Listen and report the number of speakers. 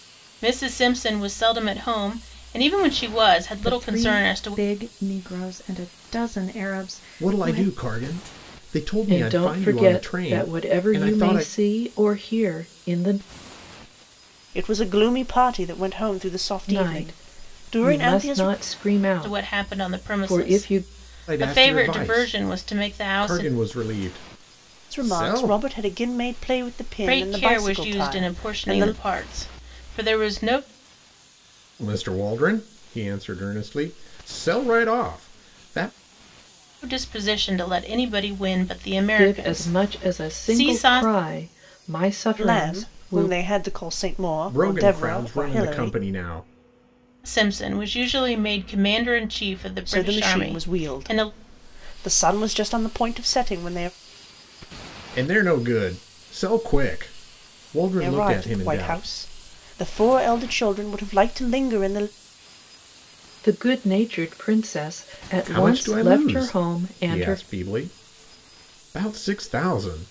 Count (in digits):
5